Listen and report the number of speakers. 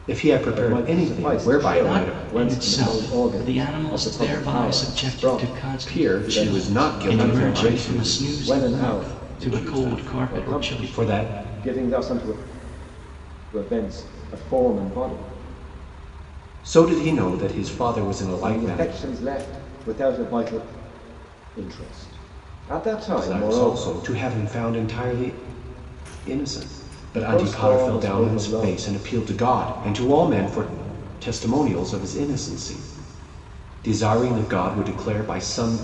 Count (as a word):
three